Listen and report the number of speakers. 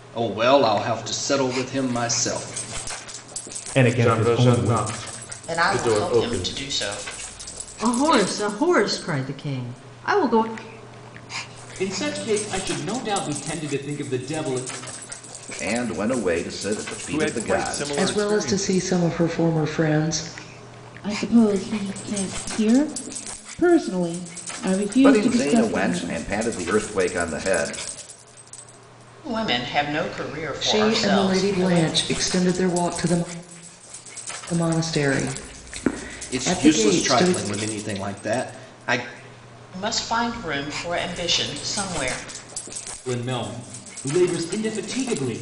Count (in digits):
10